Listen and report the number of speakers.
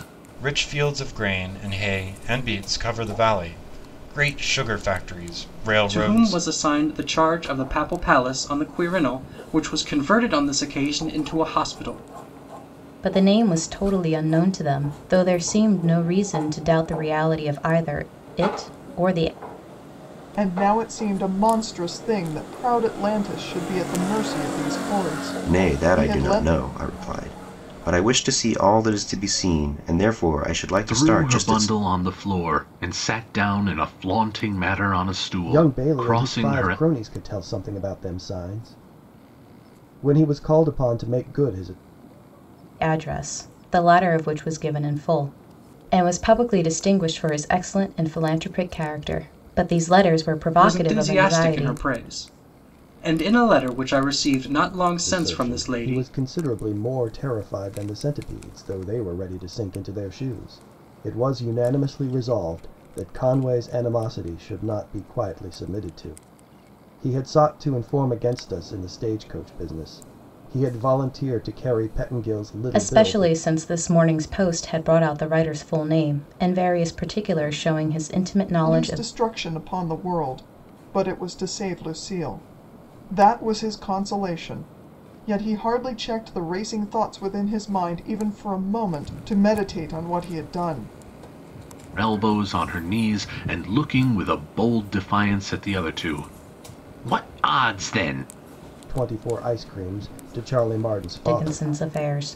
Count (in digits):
7